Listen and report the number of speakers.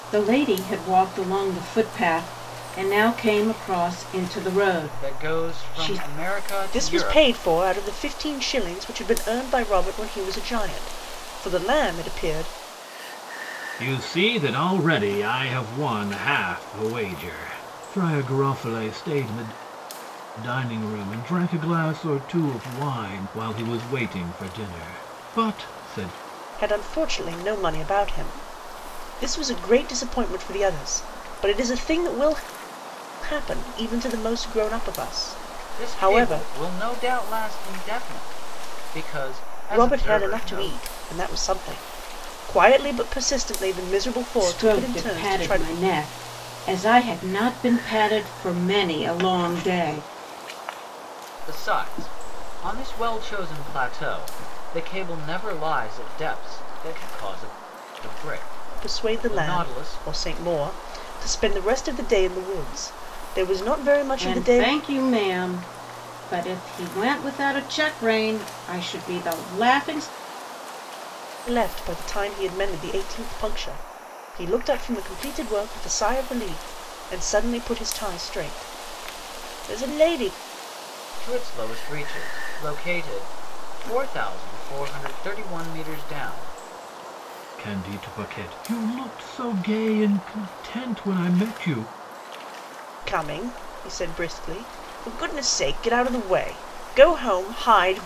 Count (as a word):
four